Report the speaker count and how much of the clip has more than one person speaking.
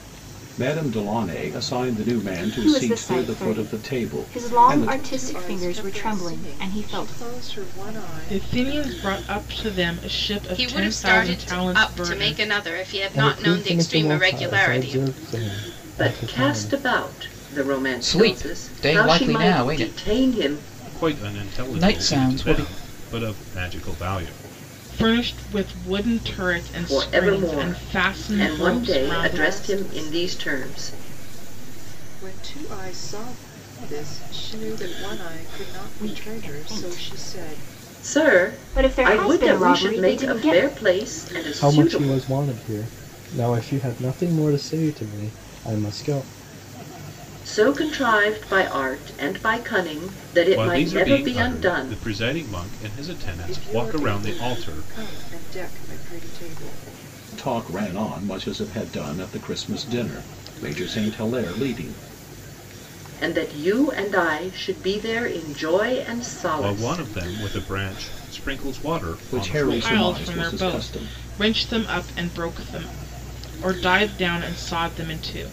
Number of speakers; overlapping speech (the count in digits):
9, about 39%